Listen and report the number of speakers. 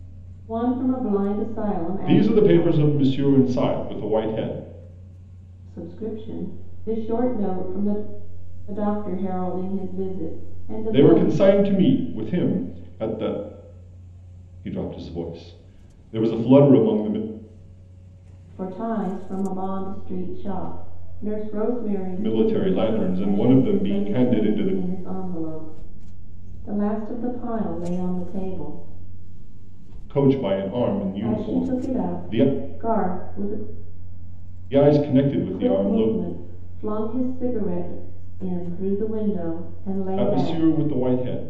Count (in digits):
2